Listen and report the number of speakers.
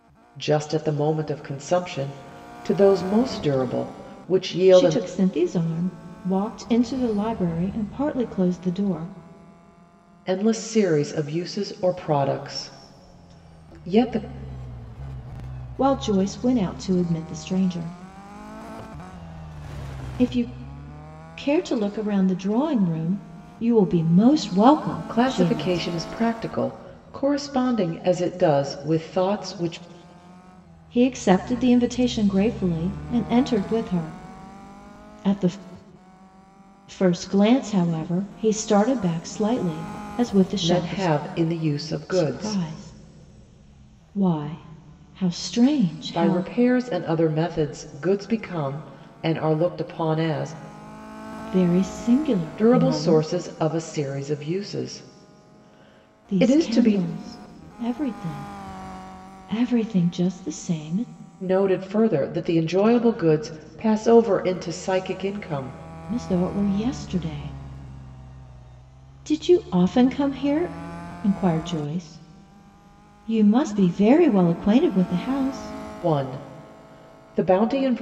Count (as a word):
two